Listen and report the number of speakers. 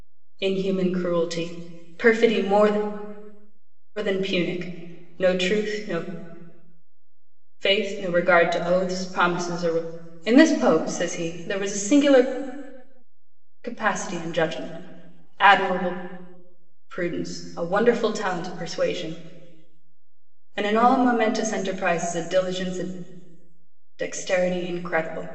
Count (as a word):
one